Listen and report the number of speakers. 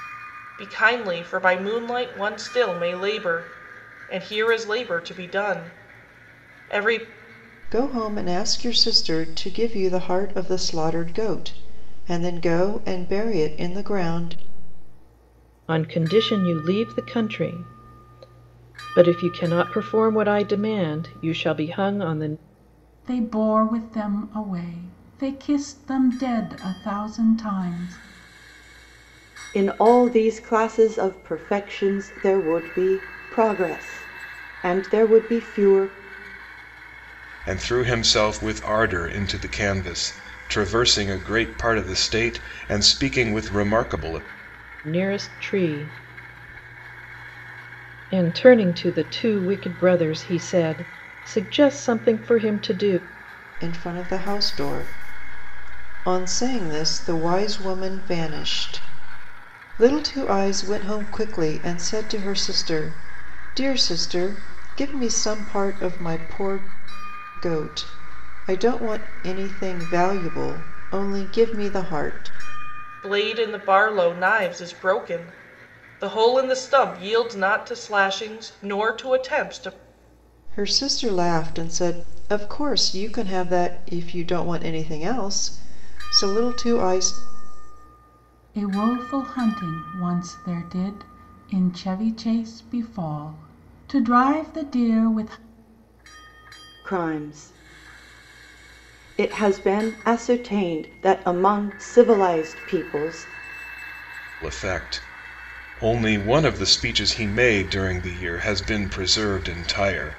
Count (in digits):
6